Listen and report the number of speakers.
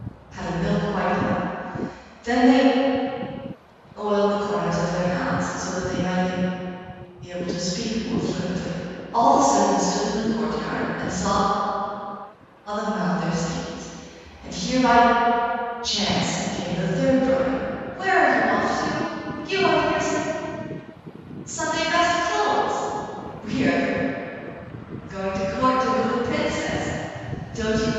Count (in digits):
1